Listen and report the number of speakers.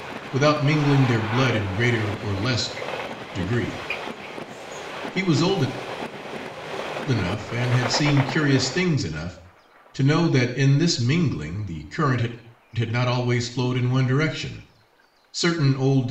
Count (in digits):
1